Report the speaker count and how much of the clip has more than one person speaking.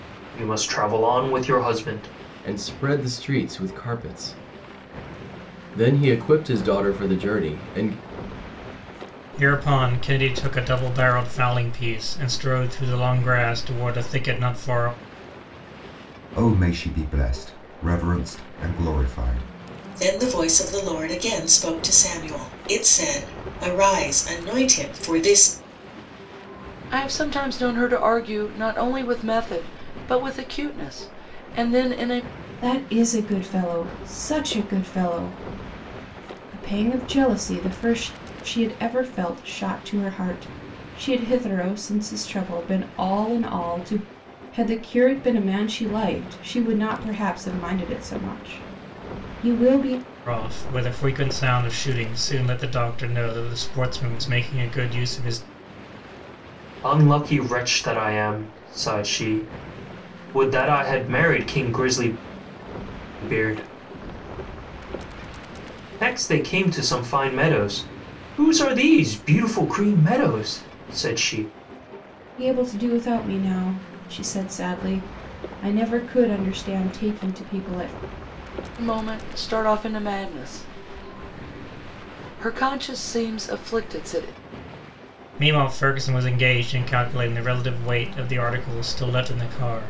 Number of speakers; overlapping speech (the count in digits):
7, no overlap